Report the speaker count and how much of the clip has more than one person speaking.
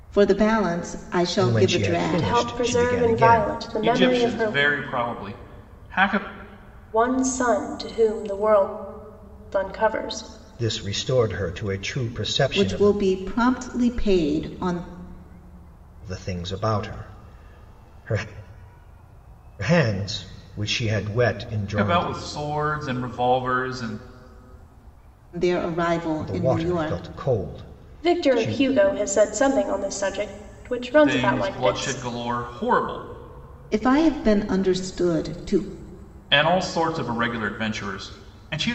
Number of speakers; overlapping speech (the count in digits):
4, about 16%